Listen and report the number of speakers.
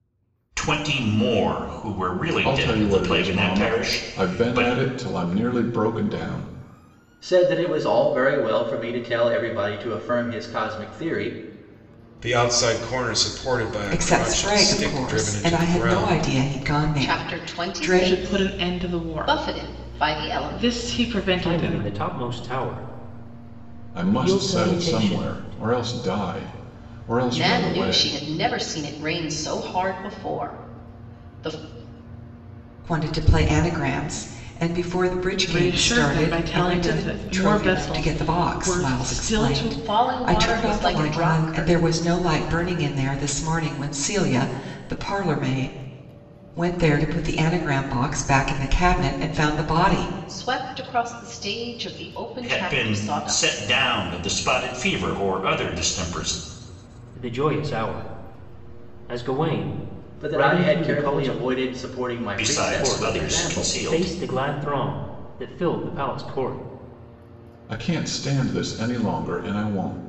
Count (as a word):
eight